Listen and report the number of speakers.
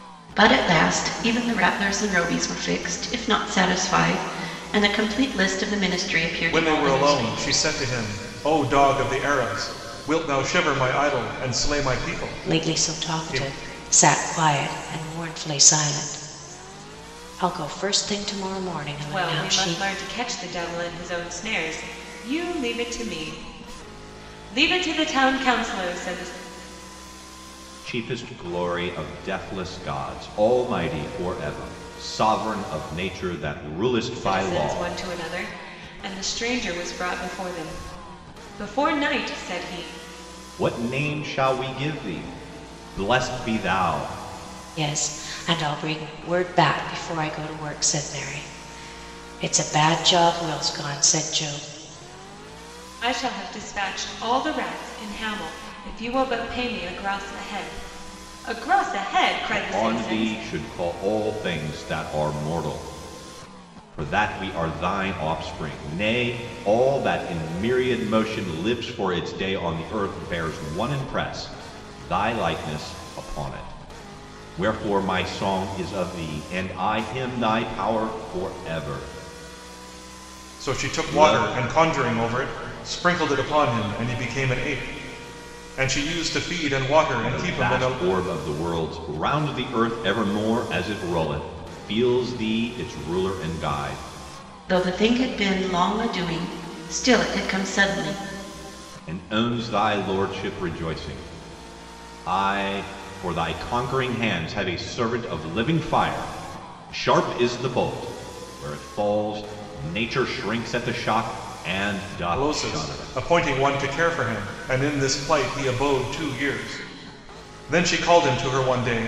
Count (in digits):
5